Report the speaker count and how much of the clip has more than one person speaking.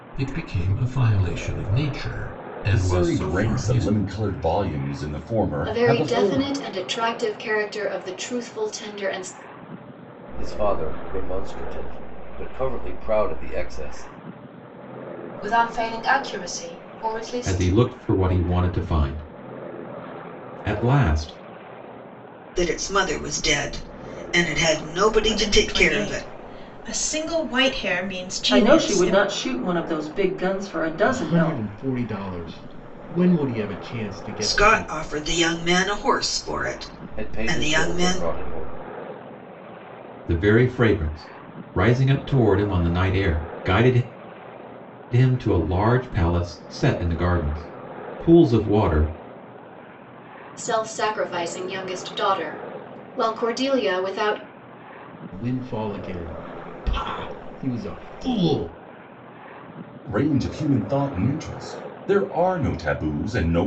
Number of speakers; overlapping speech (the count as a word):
ten, about 10%